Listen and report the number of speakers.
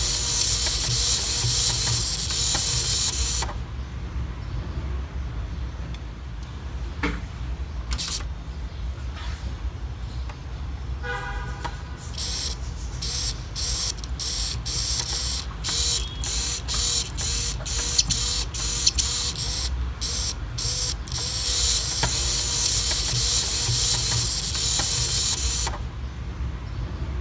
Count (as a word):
zero